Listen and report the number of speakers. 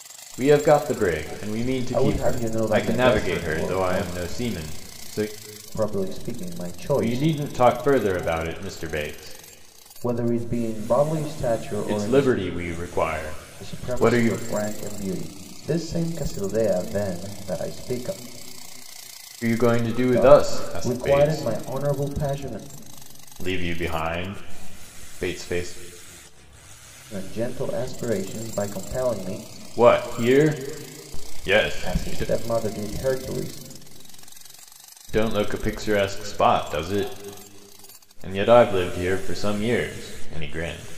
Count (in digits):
2